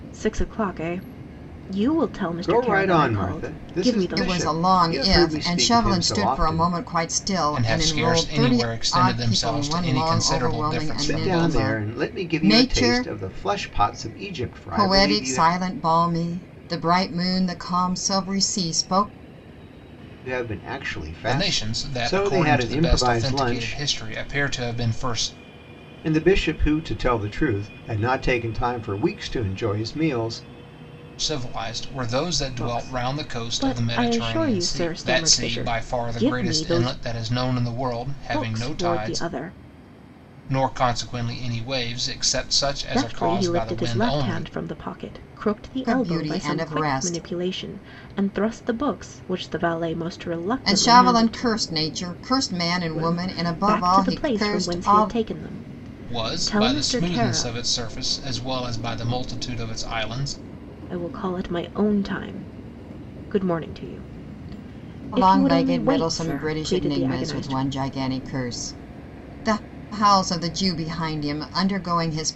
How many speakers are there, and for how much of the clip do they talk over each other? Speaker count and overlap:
4, about 40%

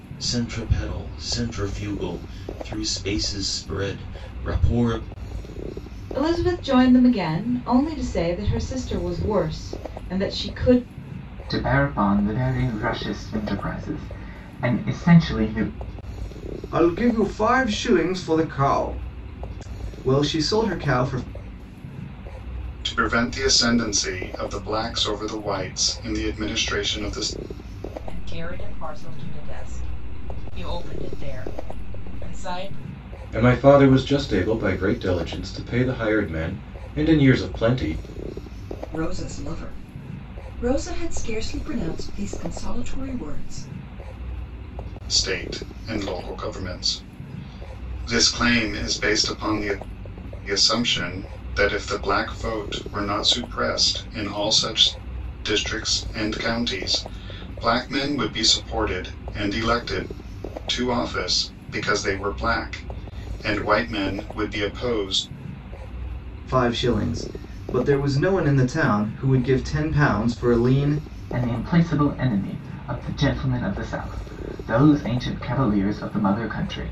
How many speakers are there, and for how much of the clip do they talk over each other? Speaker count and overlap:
8, no overlap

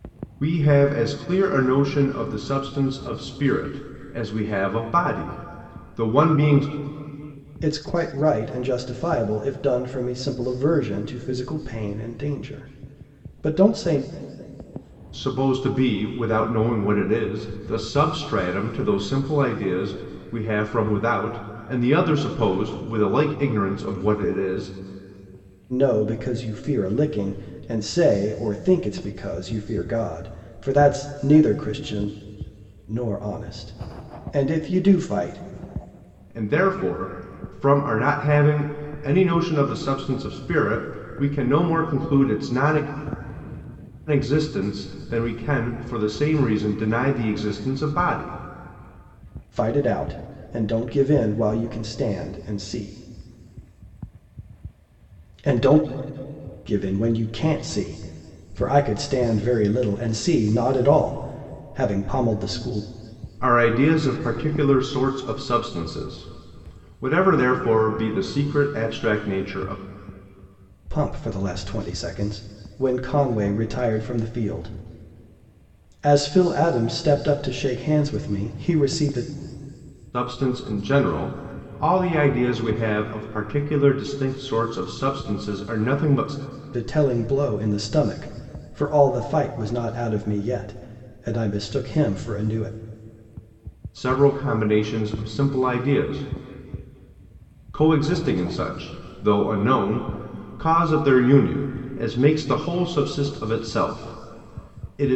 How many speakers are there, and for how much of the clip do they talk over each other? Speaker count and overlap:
2, no overlap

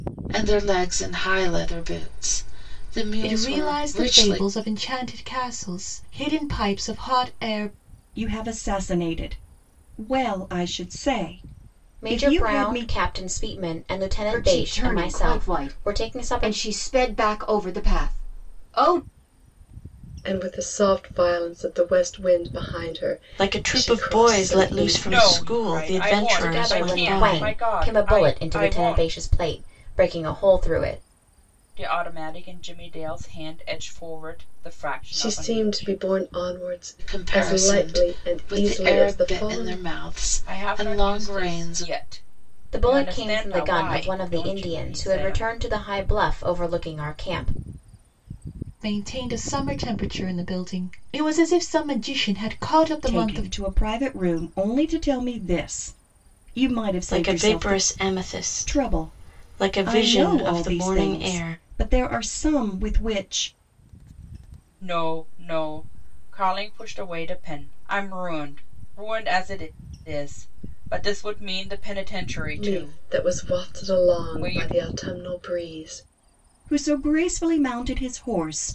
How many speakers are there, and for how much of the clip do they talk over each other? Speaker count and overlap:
8, about 31%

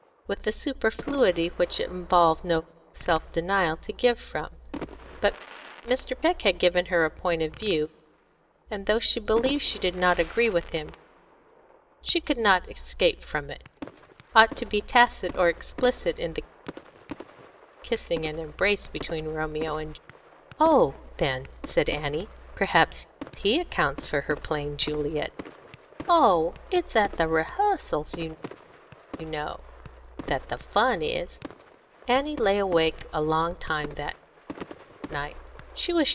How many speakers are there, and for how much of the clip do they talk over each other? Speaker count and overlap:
1, no overlap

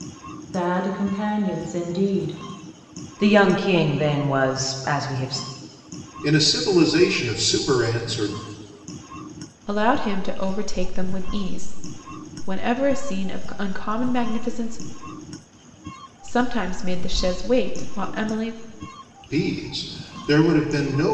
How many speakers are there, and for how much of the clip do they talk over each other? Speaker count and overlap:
4, no overlap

